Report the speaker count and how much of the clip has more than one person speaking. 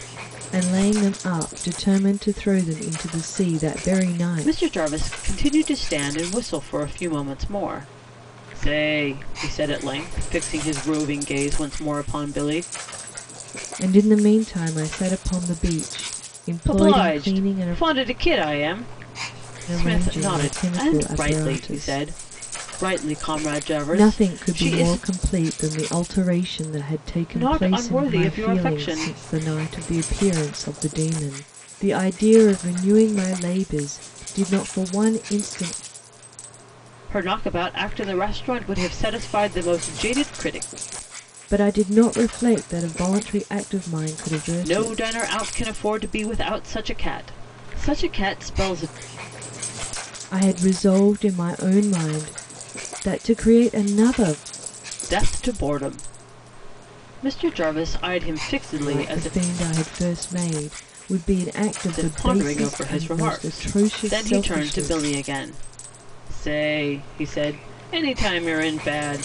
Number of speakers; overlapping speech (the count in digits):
2, about 15%